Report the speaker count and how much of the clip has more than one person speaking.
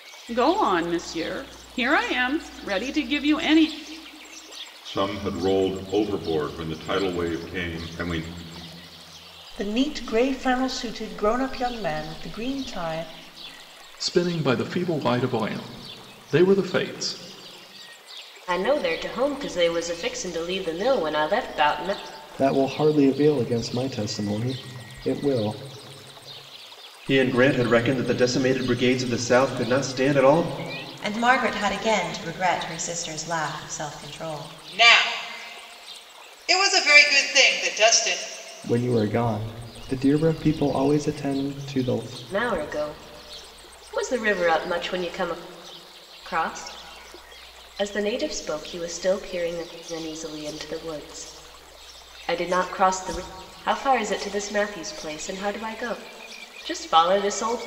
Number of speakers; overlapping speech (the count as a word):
nine, no overlap